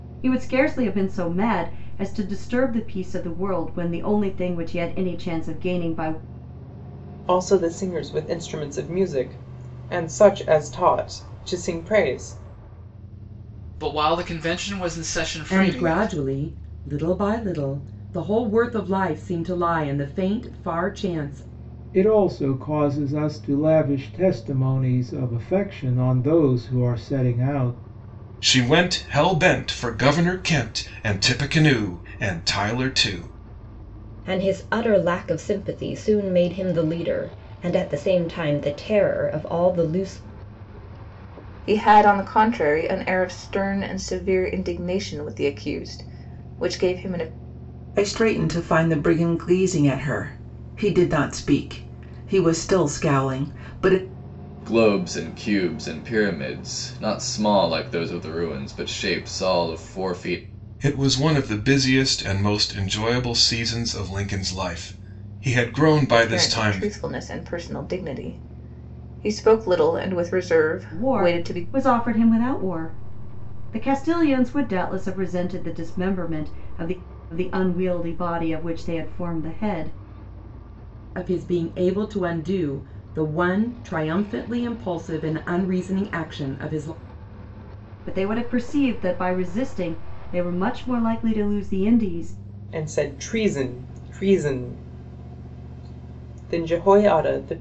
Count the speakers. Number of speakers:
ten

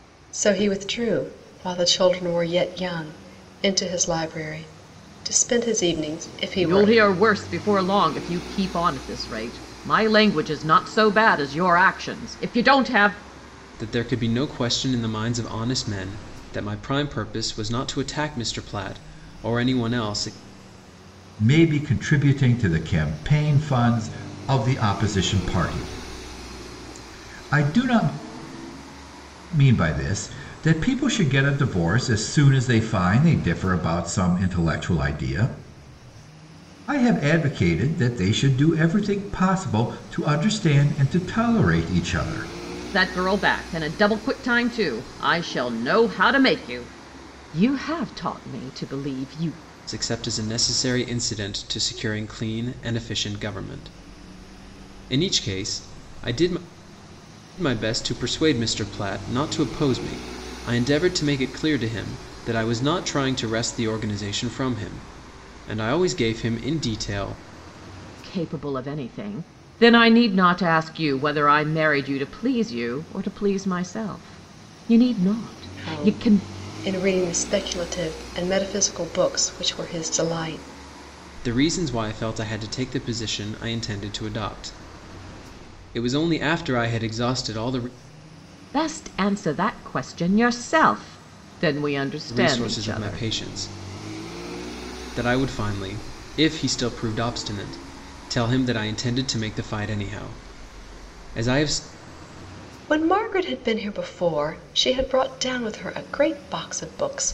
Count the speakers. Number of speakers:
four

